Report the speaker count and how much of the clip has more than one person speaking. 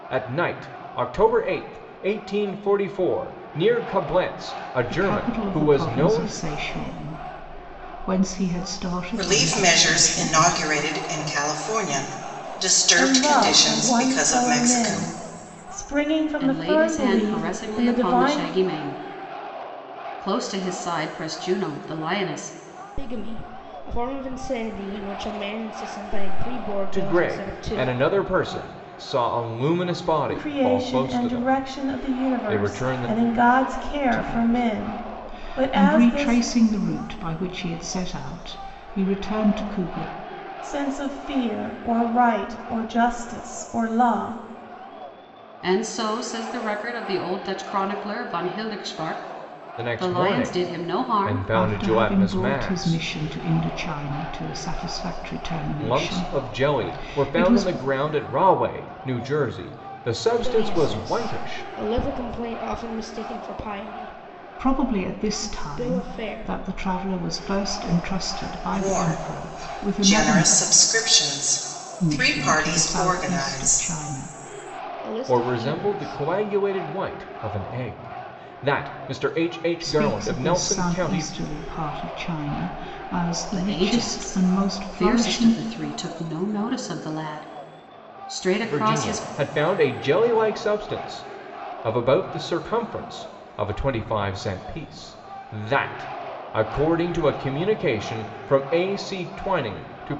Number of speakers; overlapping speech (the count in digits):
6, about 31%